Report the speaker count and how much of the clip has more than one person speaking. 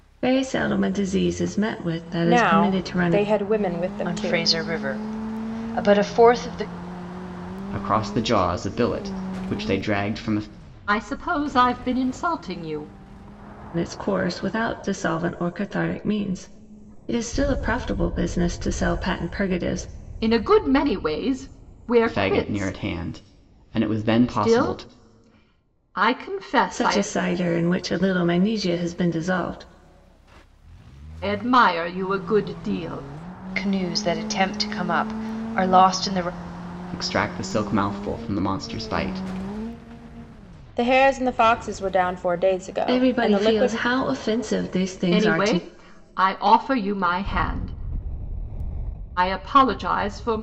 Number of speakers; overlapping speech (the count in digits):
5, about 9%